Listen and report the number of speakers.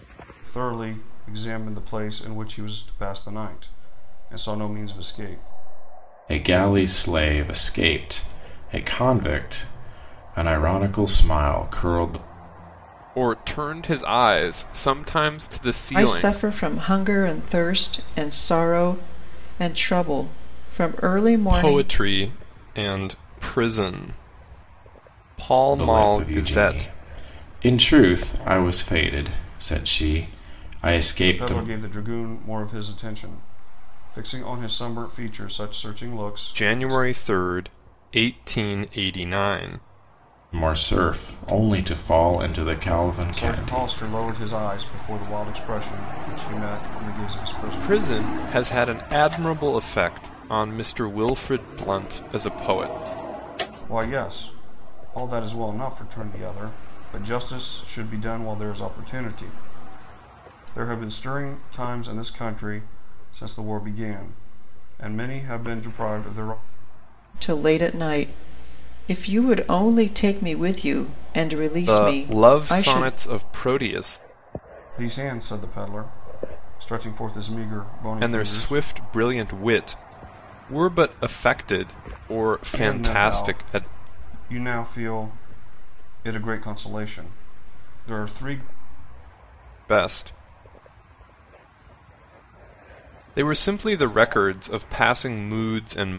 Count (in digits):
4